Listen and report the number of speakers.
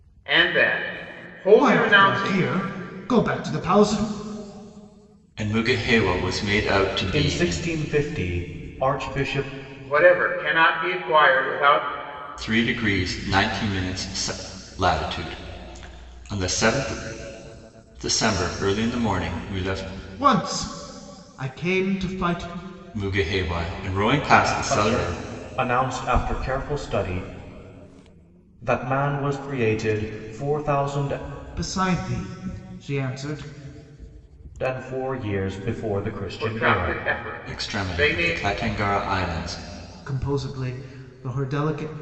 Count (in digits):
4